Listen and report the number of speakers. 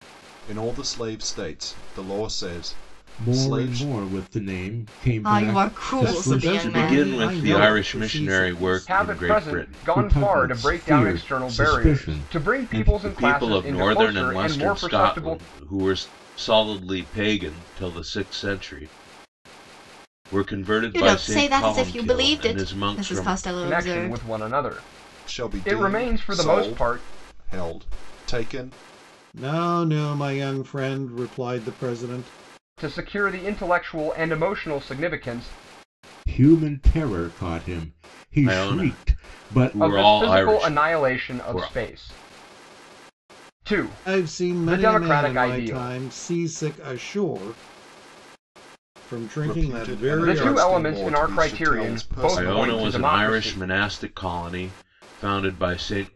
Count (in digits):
6